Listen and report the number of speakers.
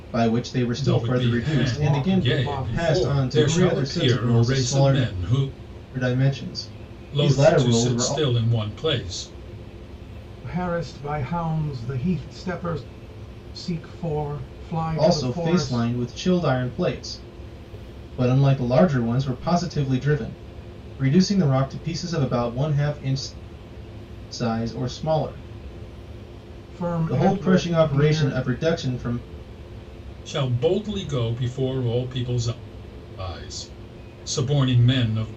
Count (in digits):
3